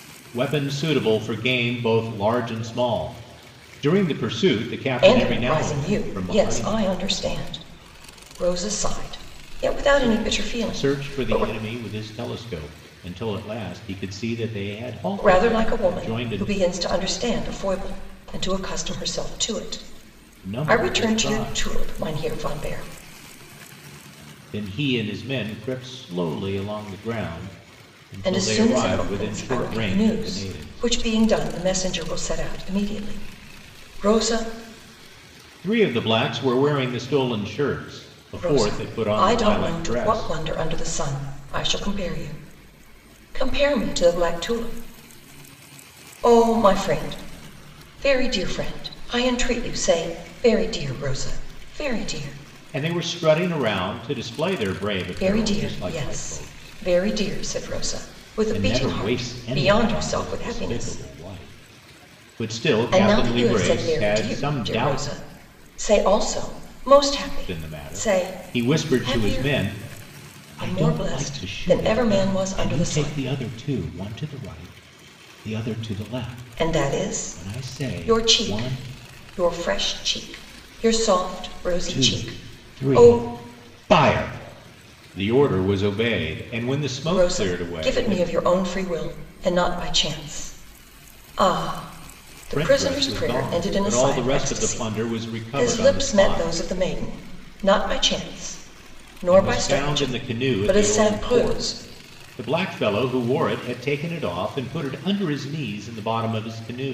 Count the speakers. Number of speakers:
2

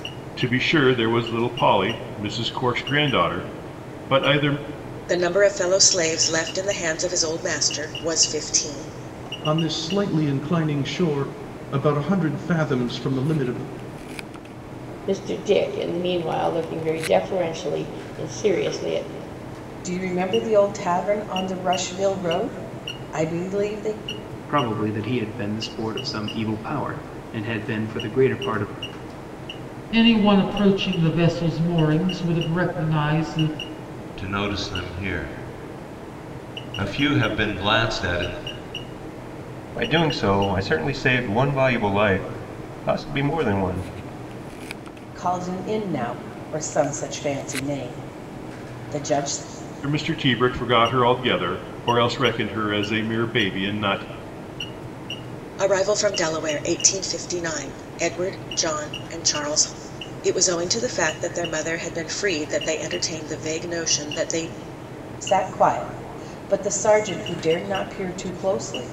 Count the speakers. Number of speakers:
9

